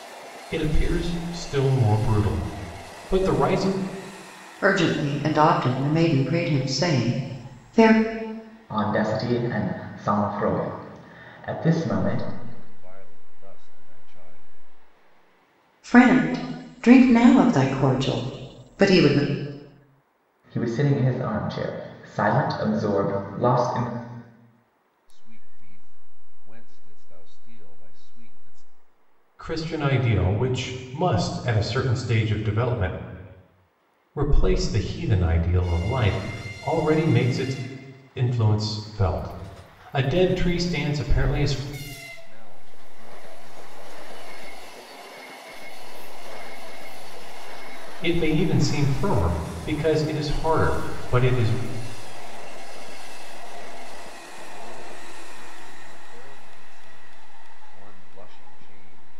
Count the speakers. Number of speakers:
4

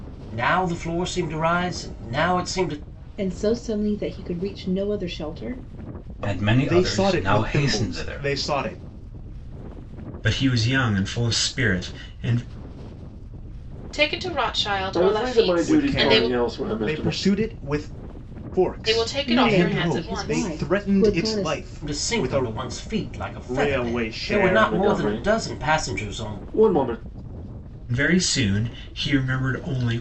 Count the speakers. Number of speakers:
7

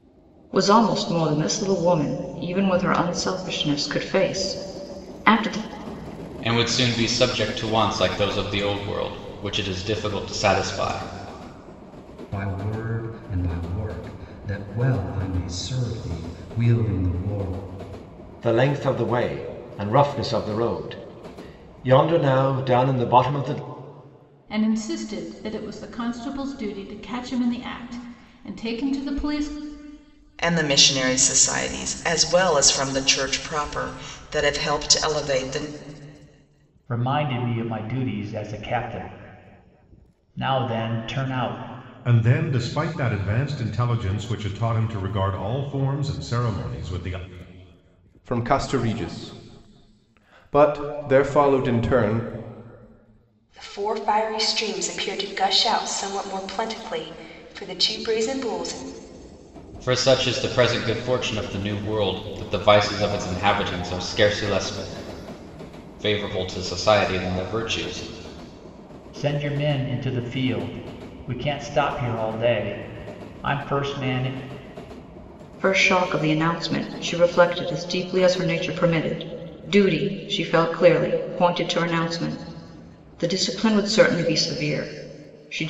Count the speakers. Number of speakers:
10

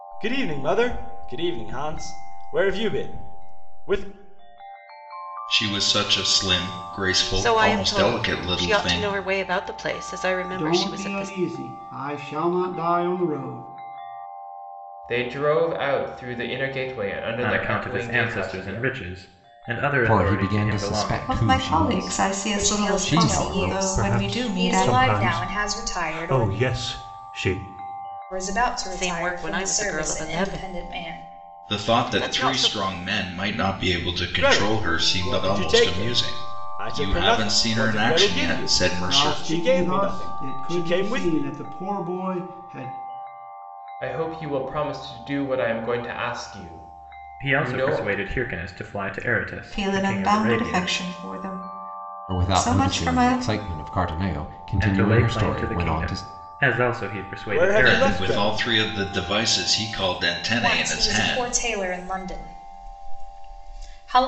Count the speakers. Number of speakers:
10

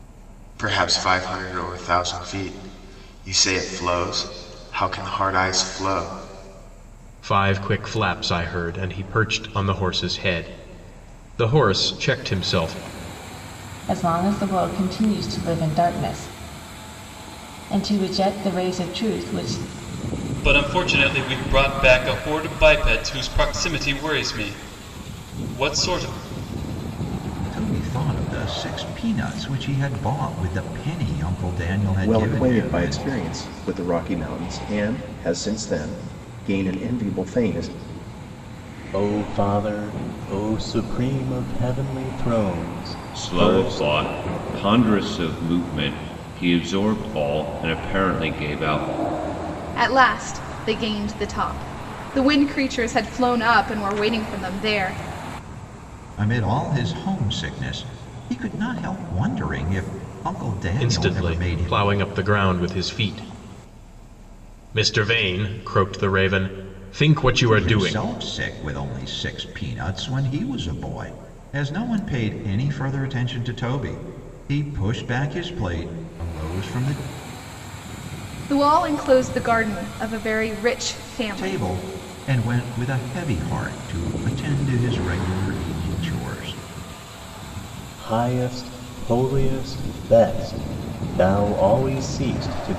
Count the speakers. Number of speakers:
9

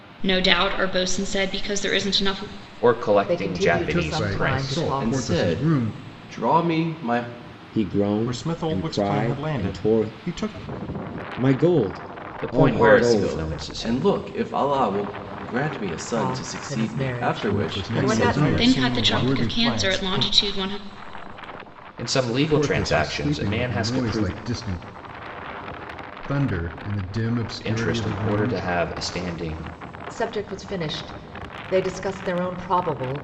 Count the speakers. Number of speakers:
7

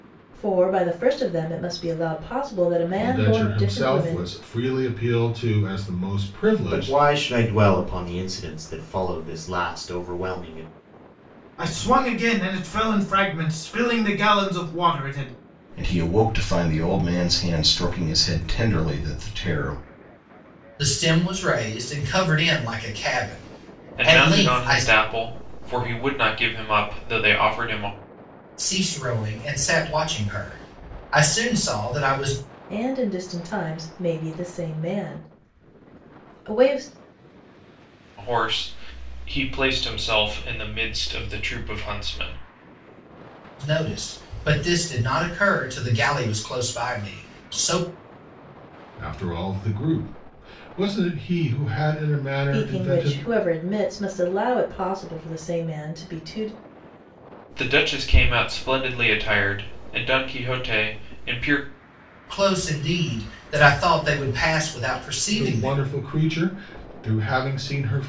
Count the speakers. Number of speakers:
7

